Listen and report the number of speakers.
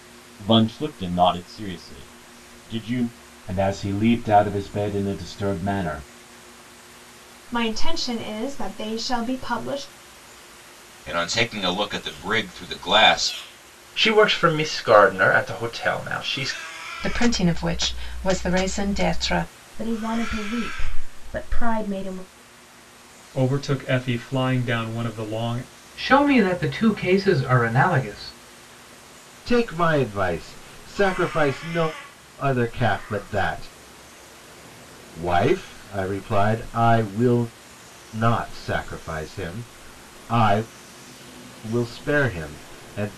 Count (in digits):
10